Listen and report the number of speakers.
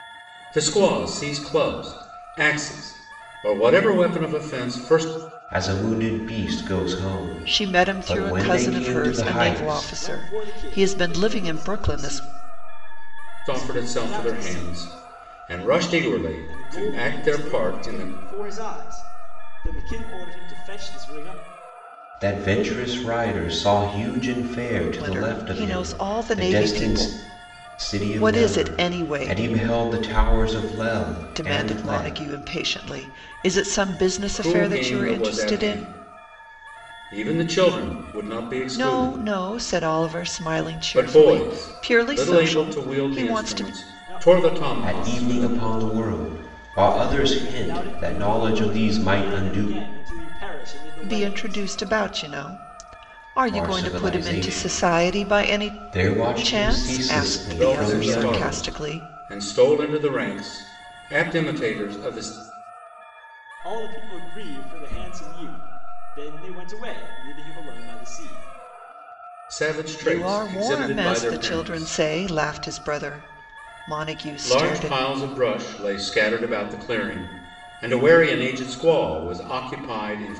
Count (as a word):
four